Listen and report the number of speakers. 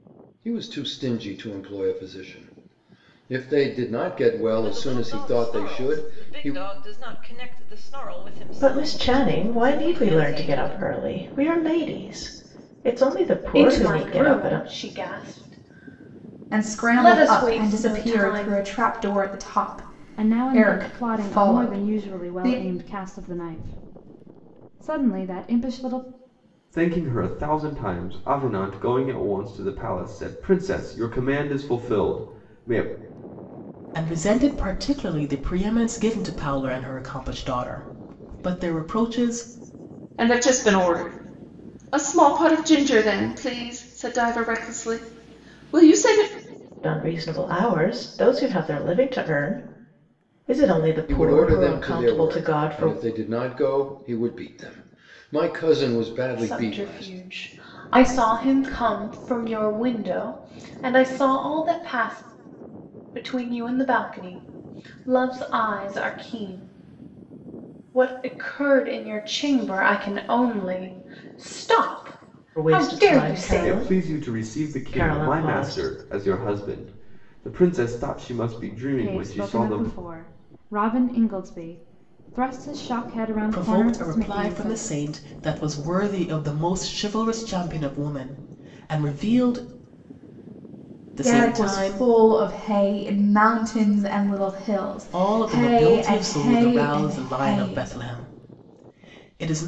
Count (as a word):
nine